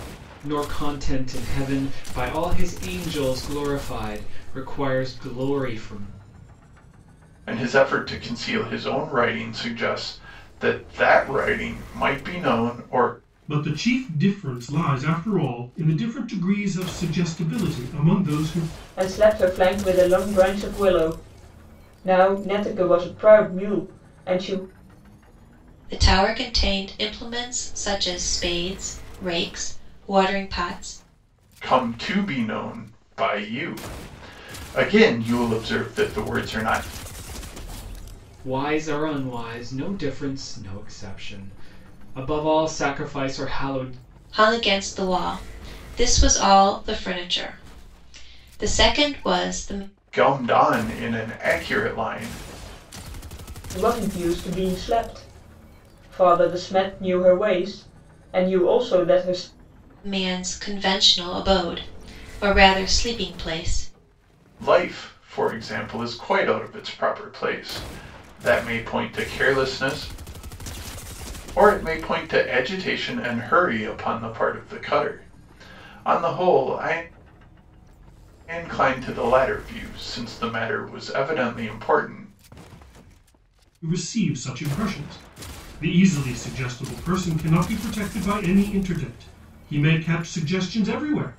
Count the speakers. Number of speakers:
5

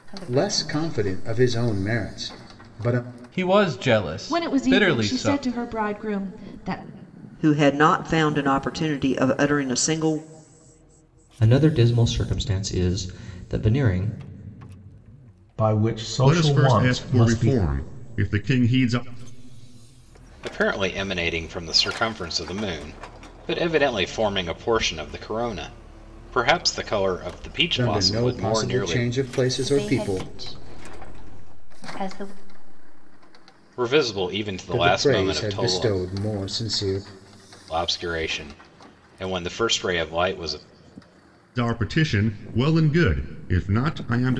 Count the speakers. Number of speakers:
9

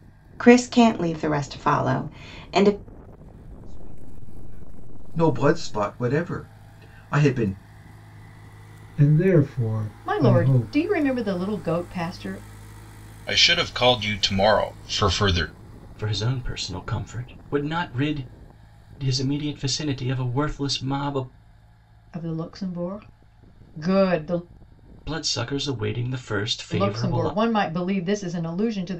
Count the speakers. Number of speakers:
7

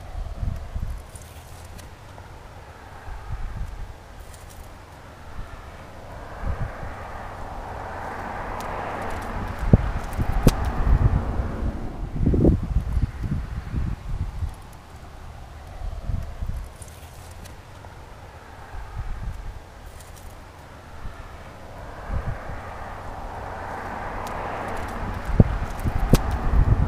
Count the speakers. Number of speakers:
0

